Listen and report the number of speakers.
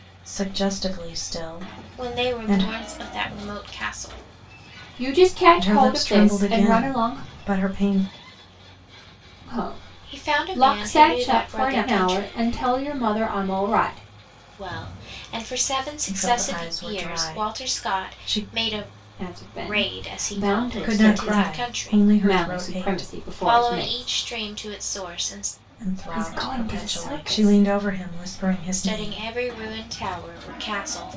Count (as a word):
three